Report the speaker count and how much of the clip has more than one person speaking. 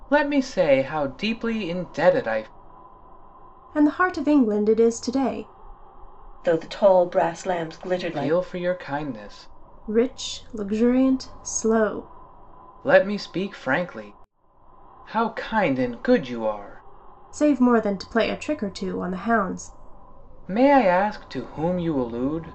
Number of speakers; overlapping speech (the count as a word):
three, about 2%